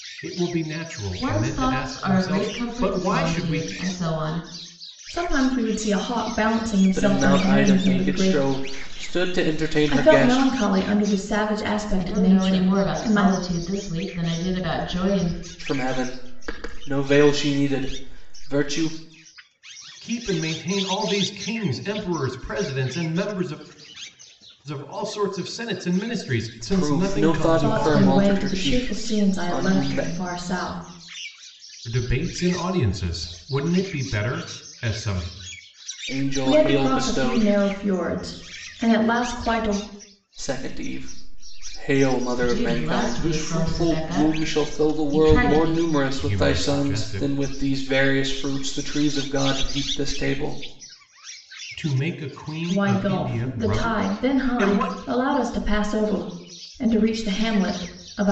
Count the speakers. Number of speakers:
4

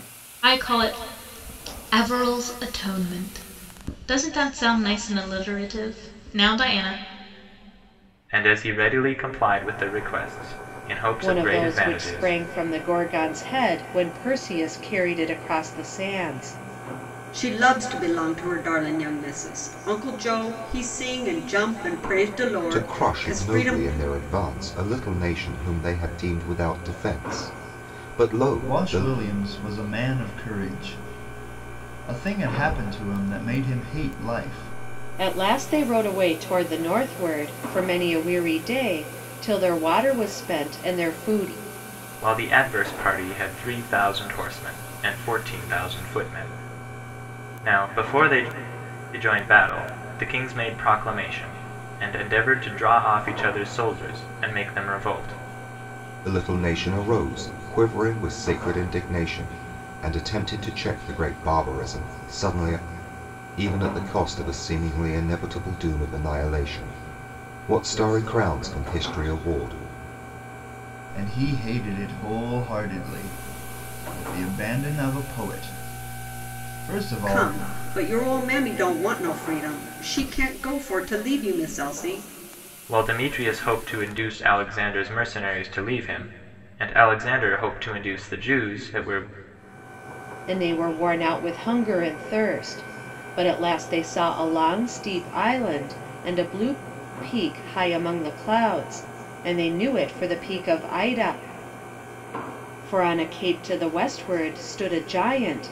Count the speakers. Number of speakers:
6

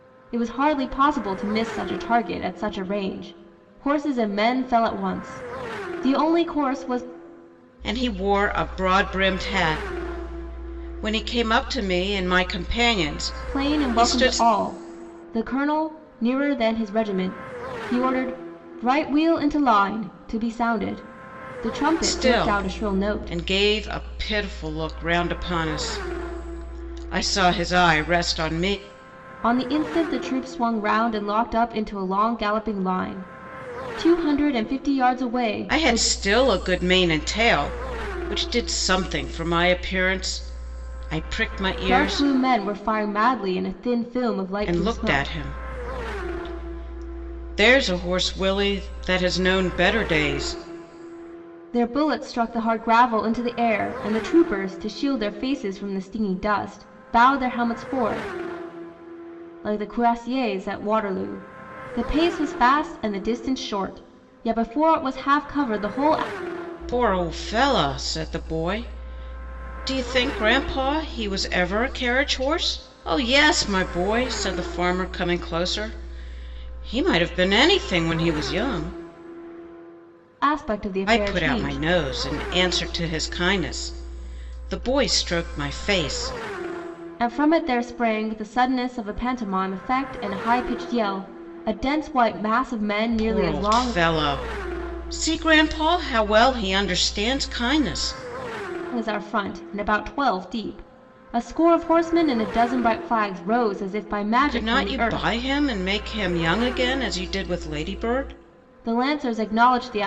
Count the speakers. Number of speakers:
2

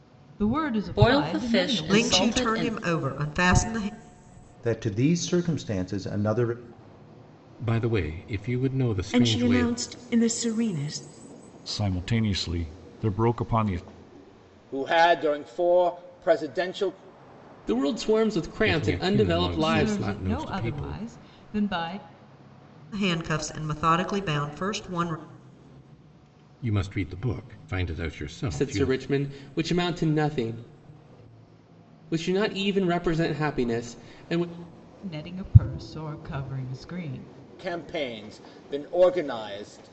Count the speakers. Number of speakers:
9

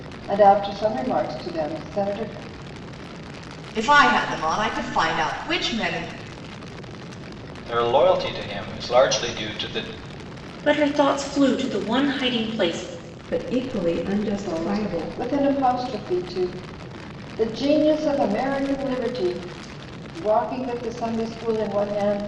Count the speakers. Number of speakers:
5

